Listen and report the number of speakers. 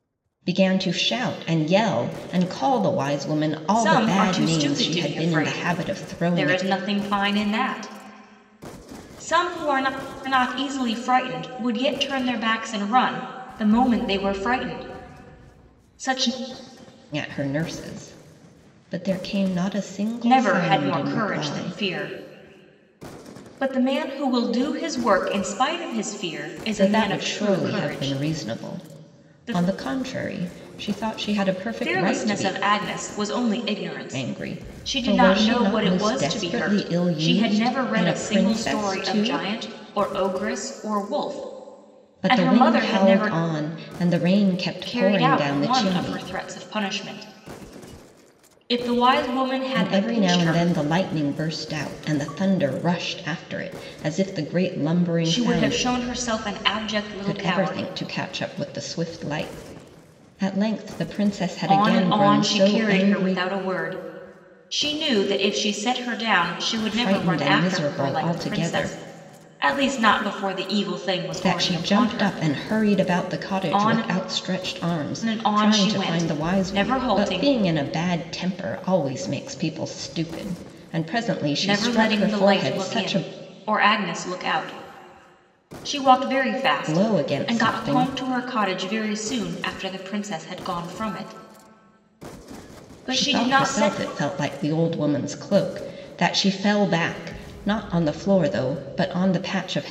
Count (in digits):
2